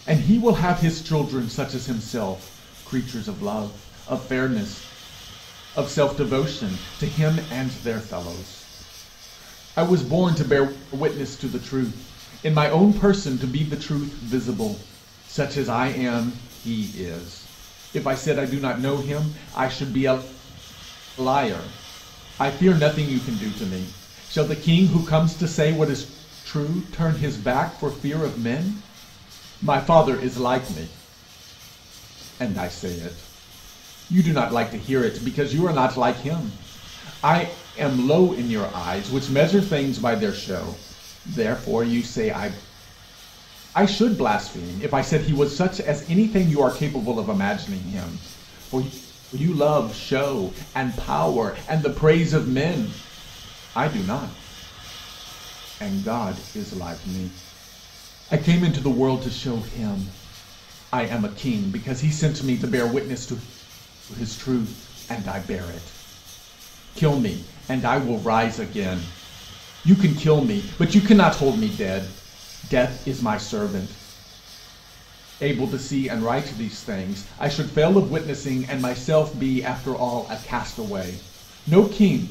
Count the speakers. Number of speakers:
1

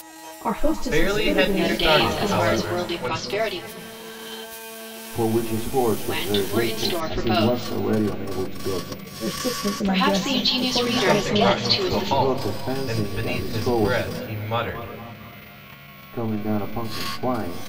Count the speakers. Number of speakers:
4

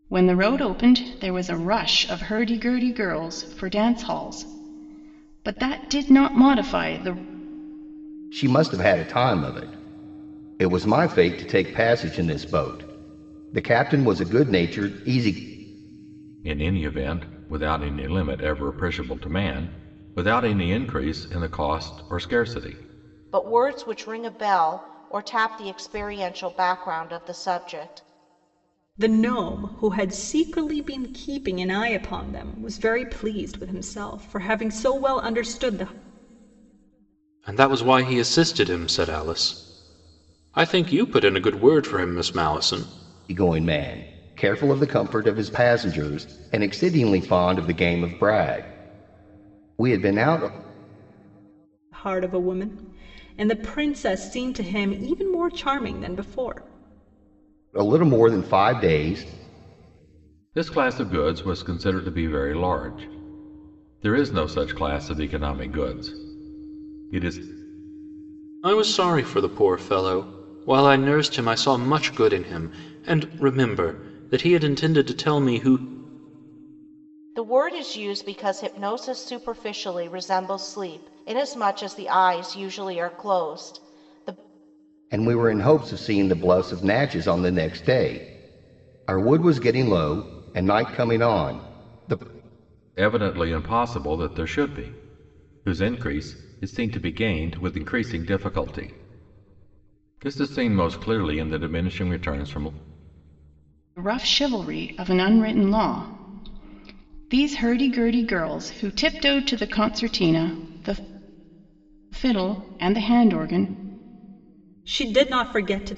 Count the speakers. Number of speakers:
6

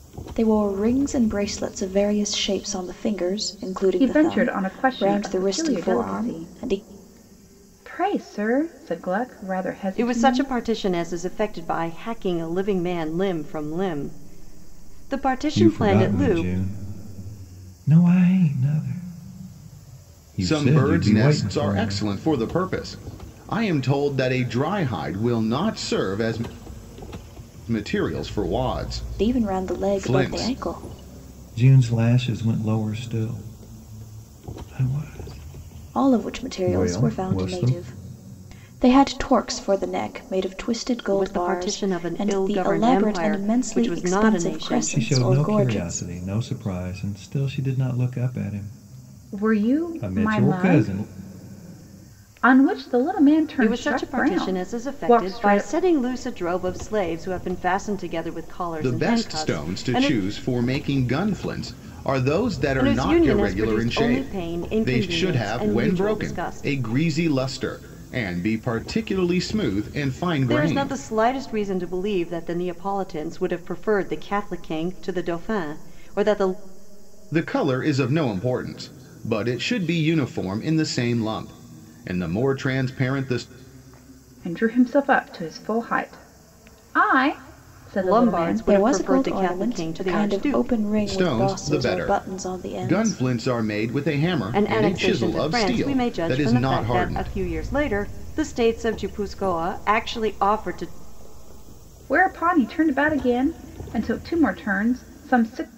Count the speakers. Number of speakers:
5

